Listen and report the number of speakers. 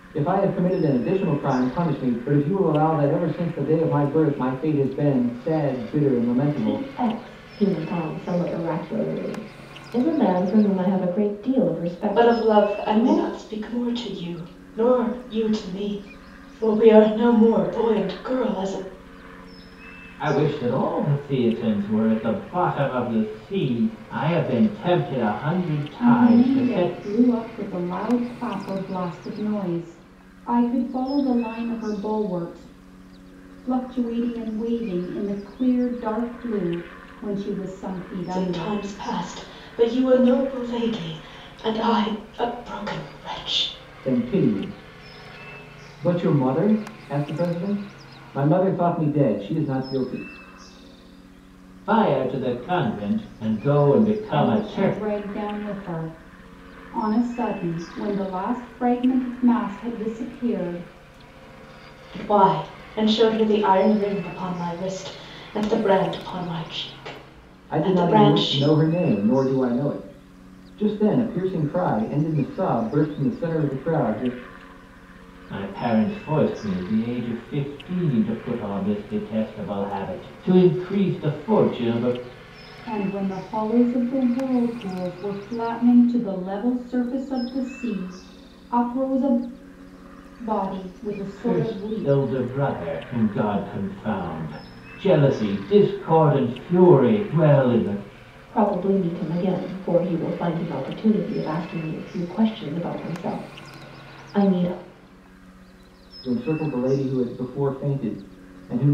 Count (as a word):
five